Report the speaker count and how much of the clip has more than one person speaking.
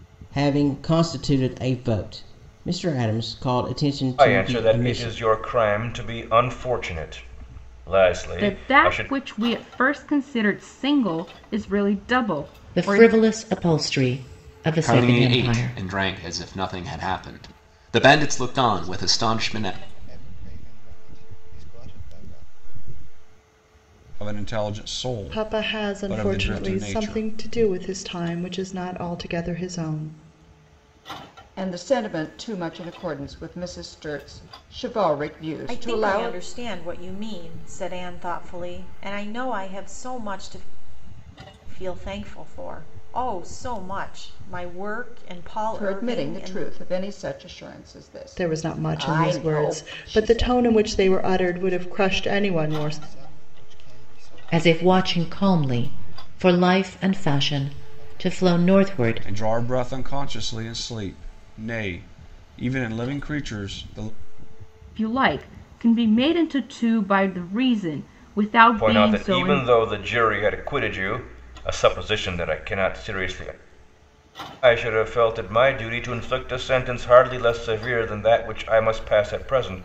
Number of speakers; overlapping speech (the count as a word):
ten, about 23%